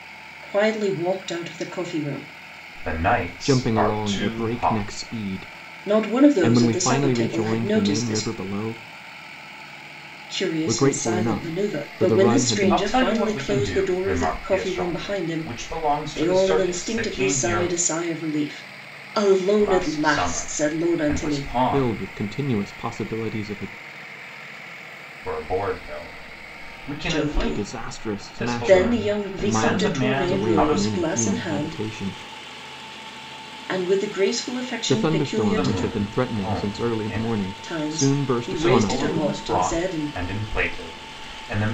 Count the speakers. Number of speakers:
three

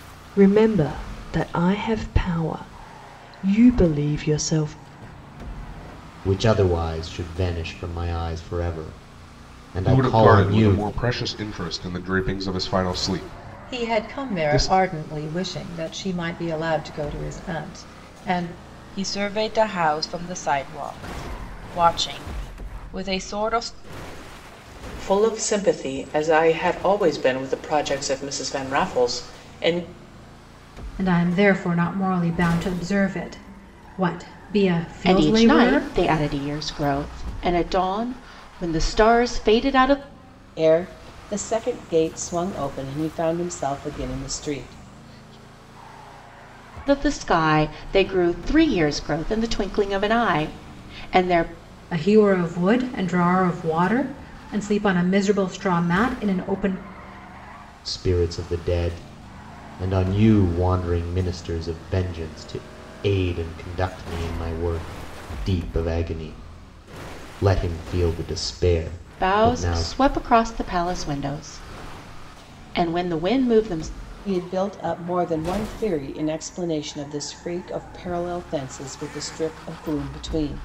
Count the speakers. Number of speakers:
nine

